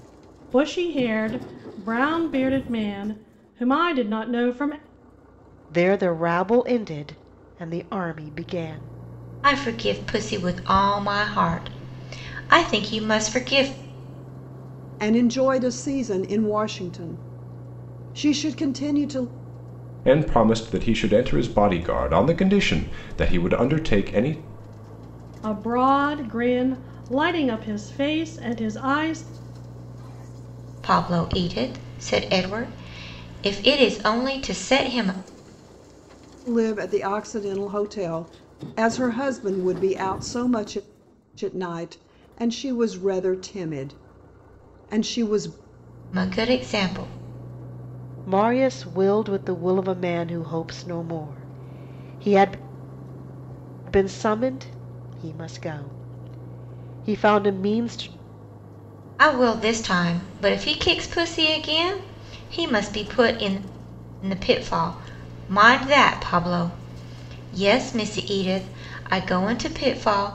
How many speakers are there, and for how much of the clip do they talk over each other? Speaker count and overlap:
5, no overlap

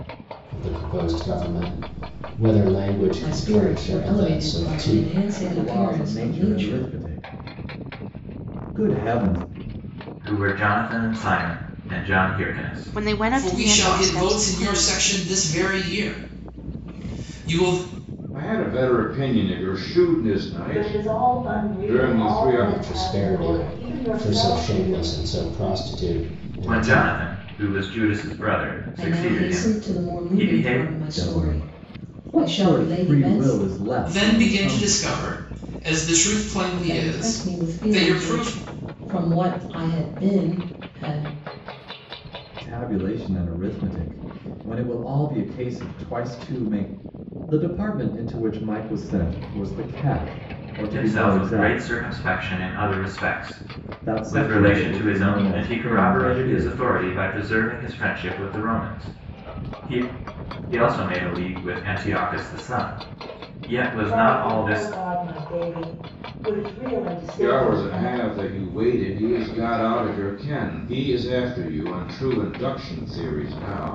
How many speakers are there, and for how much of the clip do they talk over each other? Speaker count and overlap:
8, about 31%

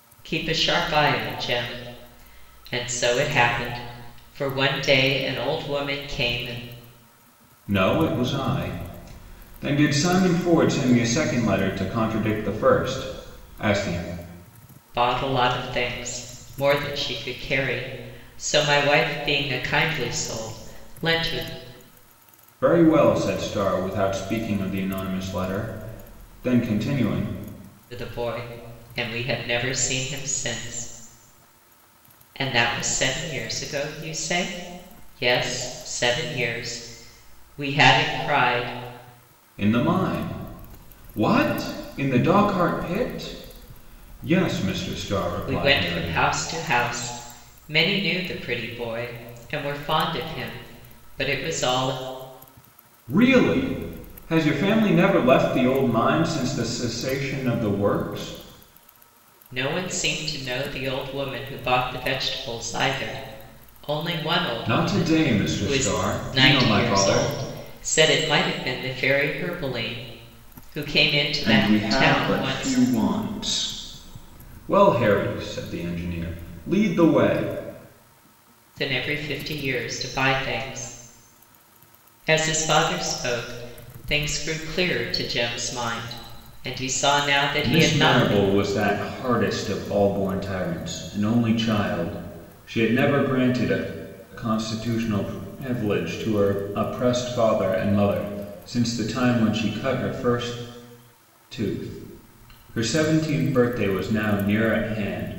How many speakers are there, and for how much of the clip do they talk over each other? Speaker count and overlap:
2, about 5%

